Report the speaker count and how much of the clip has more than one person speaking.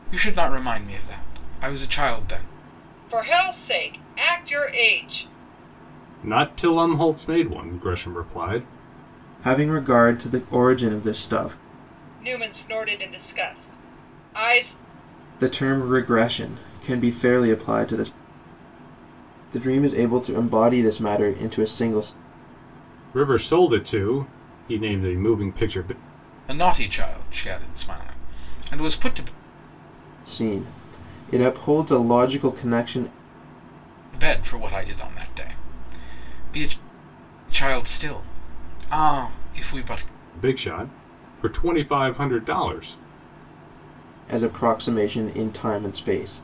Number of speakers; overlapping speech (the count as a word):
four, no overlap